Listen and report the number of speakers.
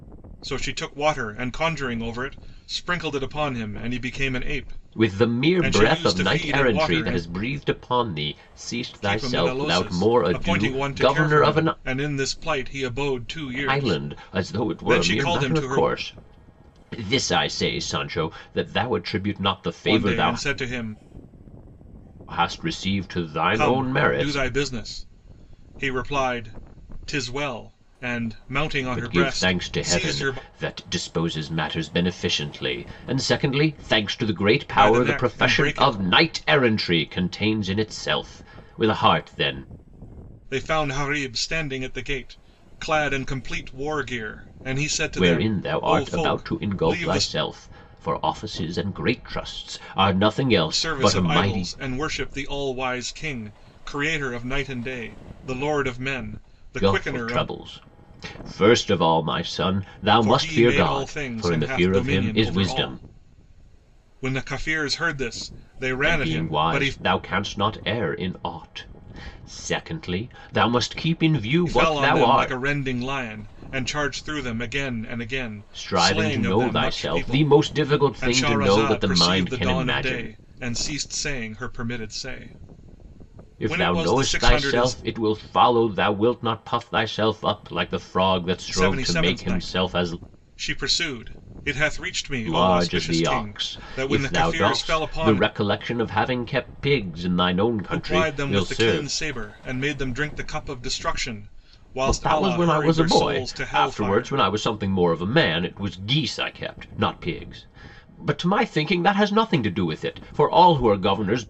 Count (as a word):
two